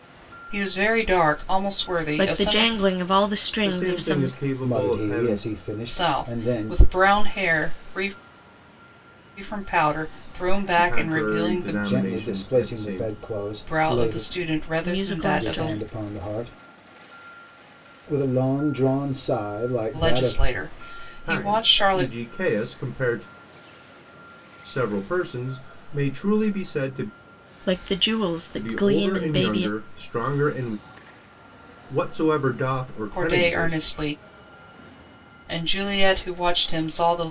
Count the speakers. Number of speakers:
4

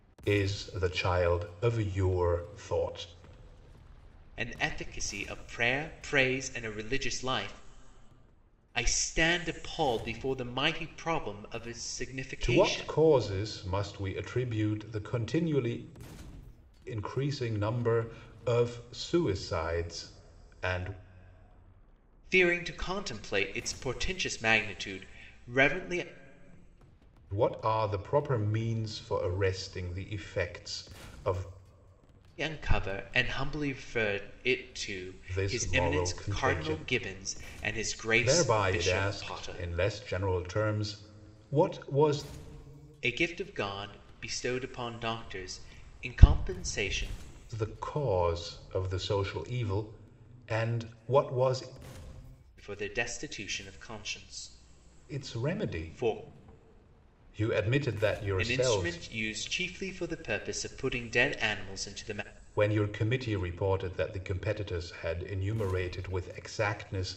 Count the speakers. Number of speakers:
2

